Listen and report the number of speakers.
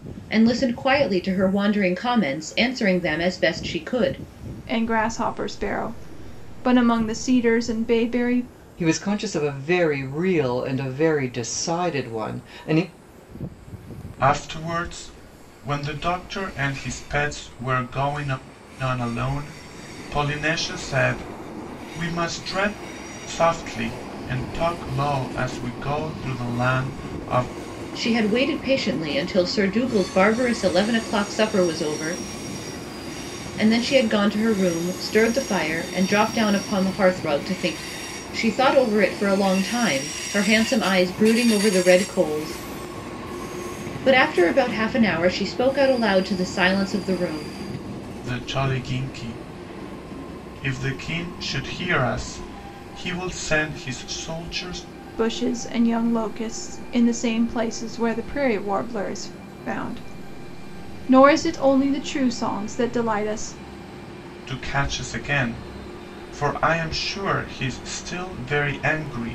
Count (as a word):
four